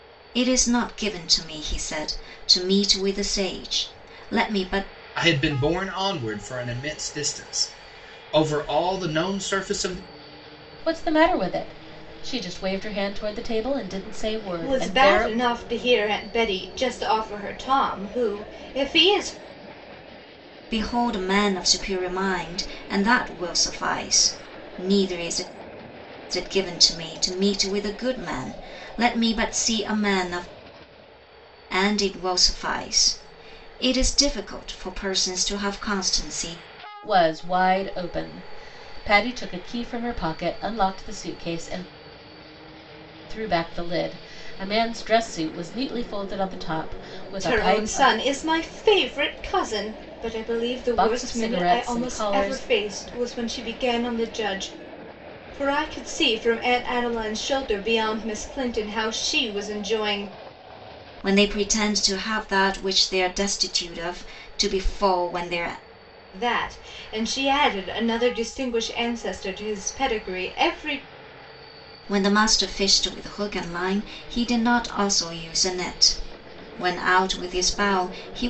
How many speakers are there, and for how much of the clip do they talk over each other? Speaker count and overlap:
4, about 4%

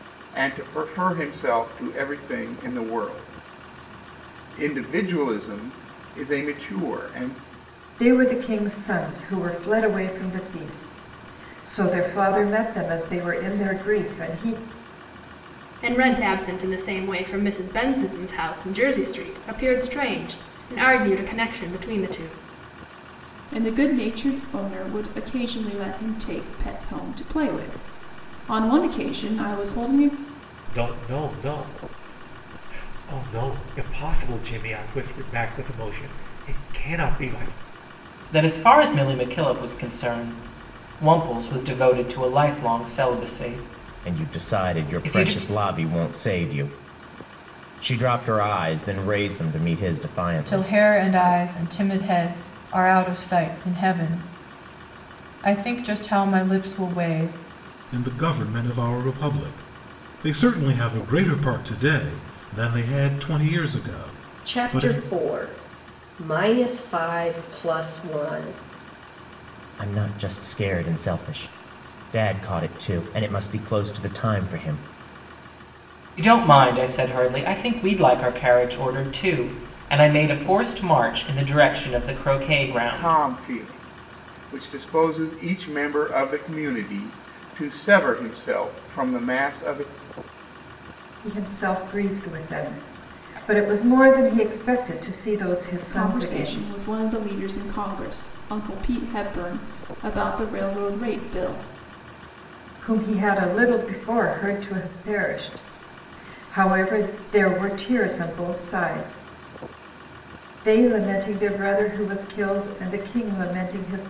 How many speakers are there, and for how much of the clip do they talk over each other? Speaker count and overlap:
10, about 3%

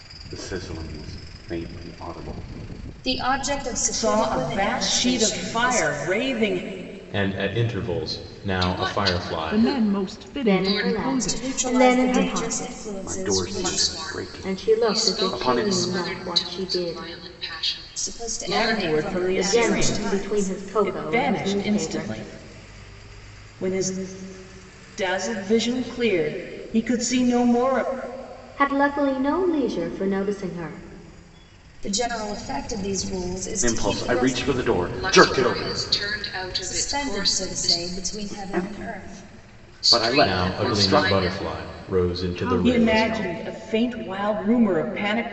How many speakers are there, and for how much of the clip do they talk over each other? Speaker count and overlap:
7, about 46%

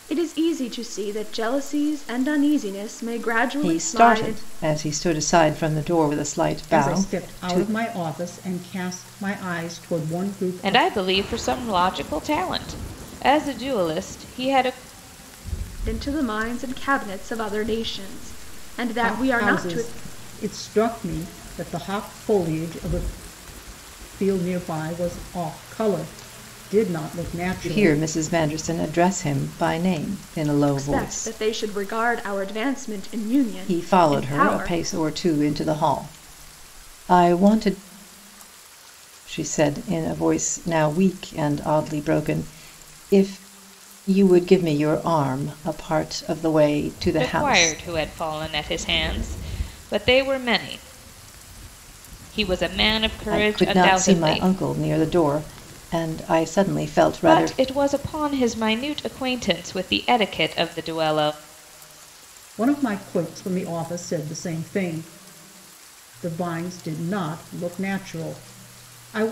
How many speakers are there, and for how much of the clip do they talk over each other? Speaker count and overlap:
4, about 11%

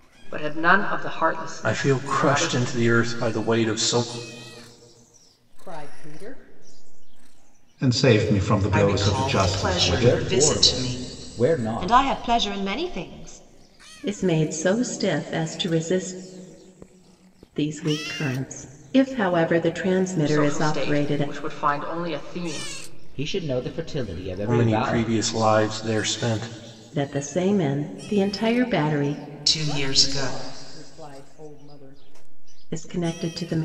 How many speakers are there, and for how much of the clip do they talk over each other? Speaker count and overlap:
8, about 18%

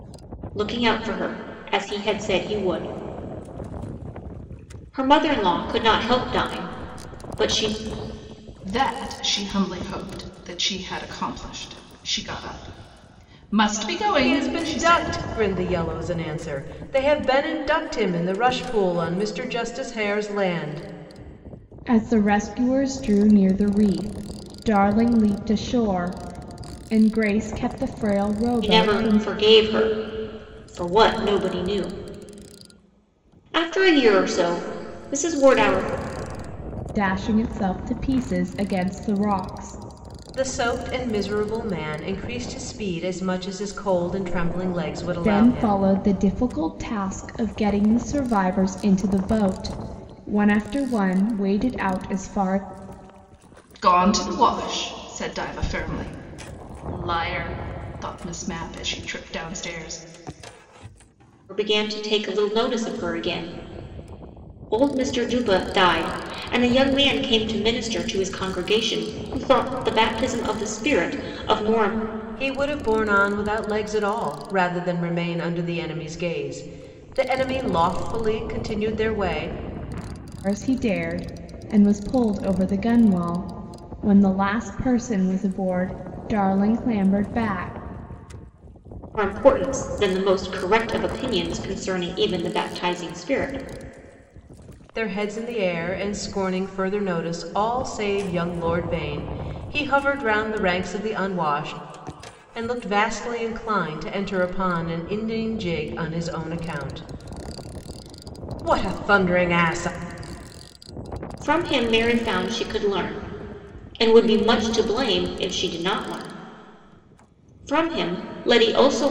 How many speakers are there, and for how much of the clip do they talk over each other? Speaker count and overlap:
4, about 2%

